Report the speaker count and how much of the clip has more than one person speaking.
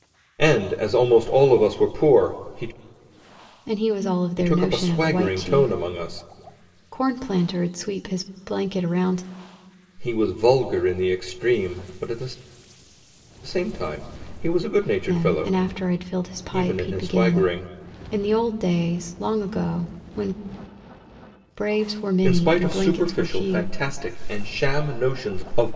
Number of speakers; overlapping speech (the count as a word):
two, about 17%